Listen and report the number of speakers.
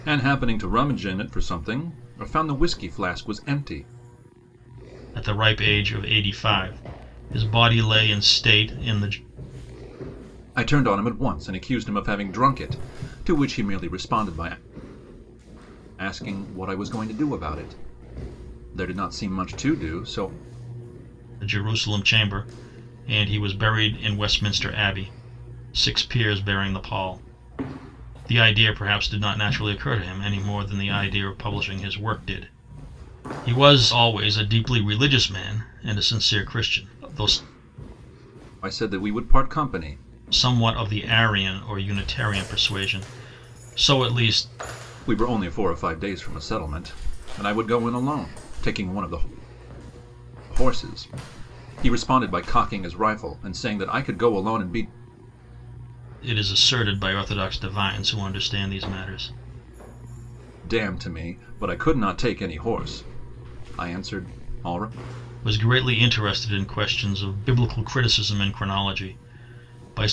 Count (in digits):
2